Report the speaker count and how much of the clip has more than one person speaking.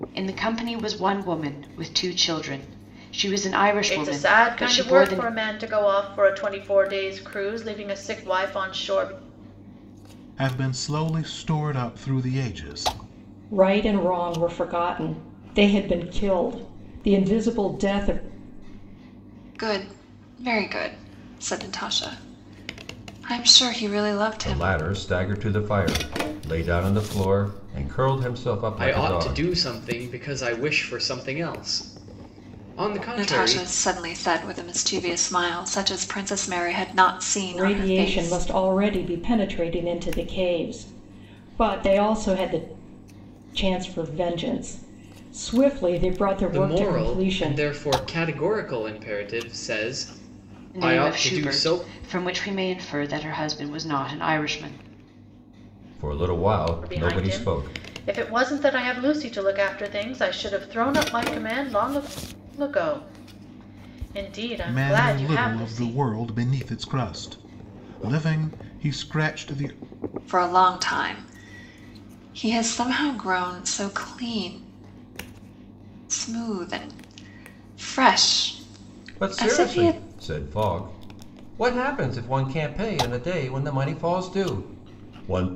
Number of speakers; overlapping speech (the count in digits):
7, about 11%